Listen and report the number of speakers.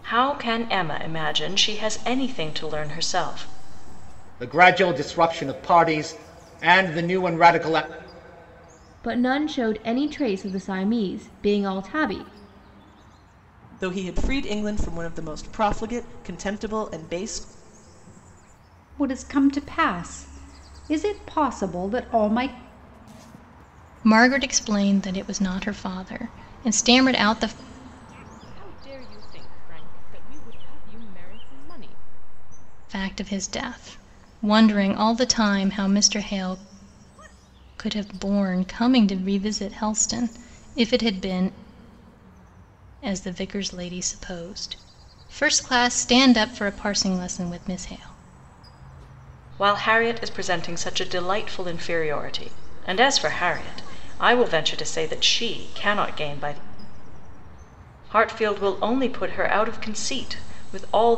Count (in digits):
7